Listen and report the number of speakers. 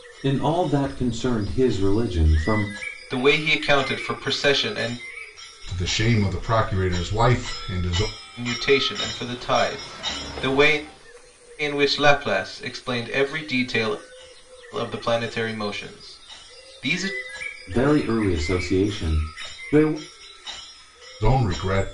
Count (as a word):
three